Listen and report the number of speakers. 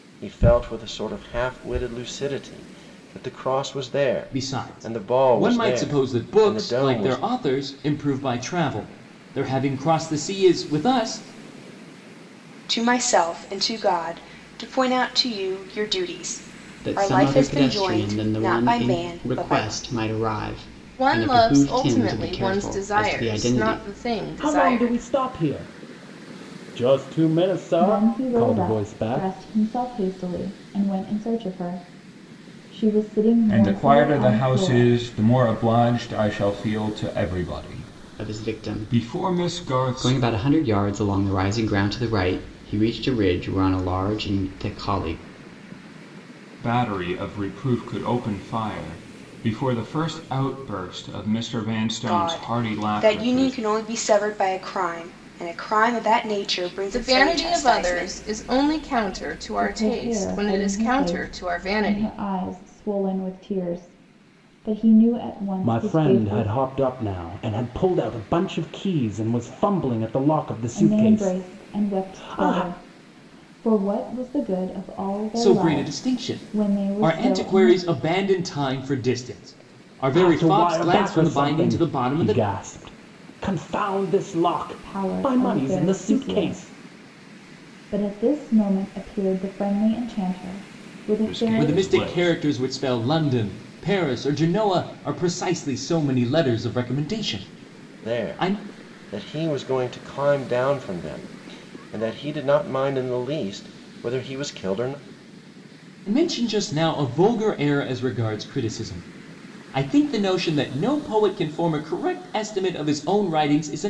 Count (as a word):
eight